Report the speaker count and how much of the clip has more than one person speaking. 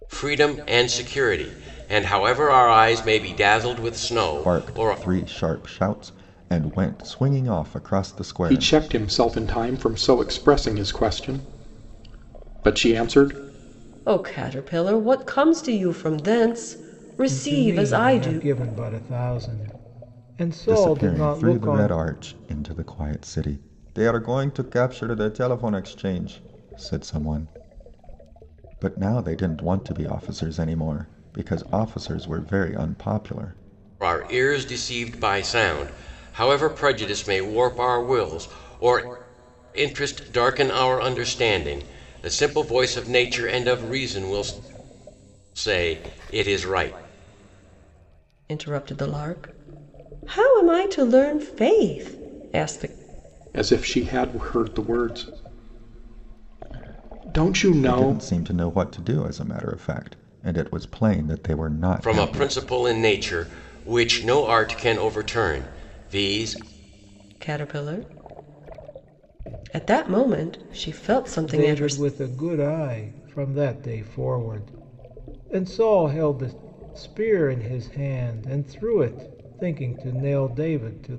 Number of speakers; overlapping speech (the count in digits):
5, about 6%